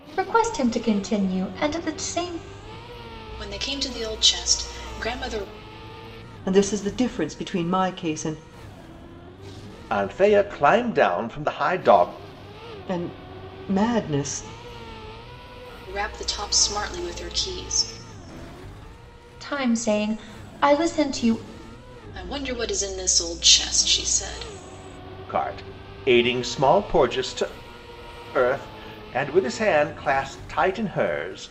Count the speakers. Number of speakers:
4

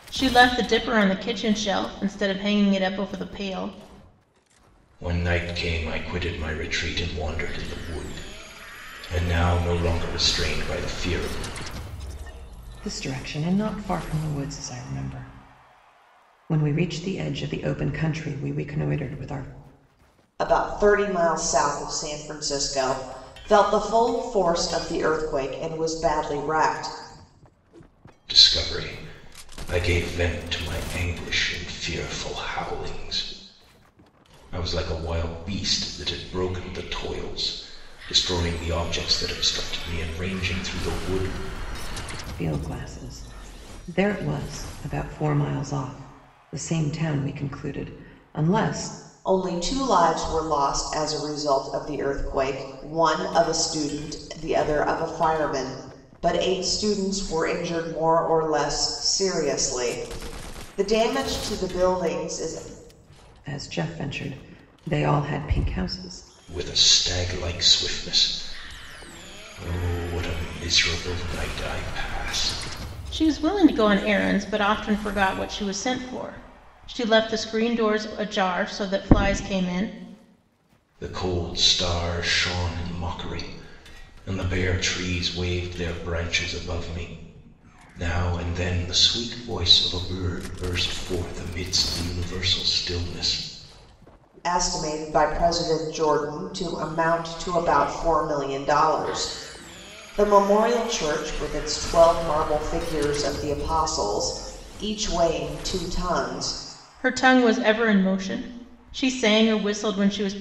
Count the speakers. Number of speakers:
4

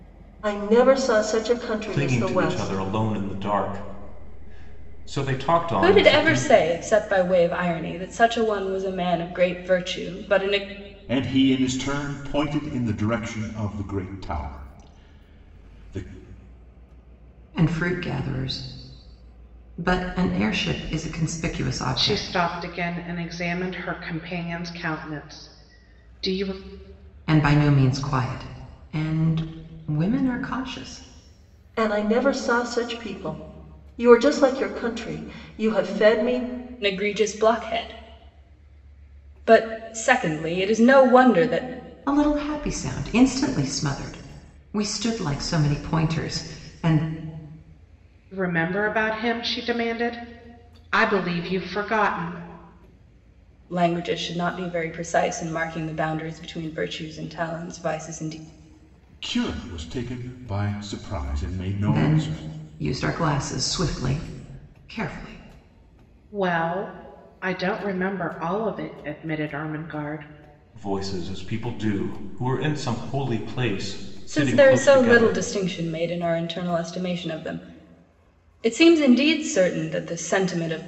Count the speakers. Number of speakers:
6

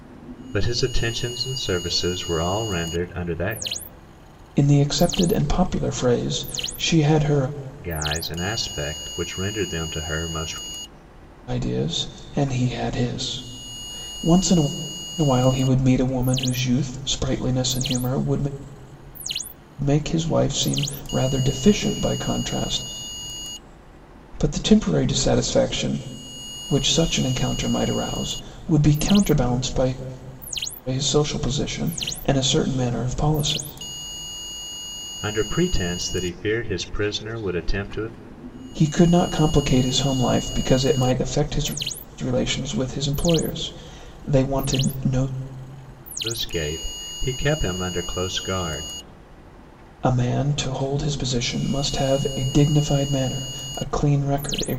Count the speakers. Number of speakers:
2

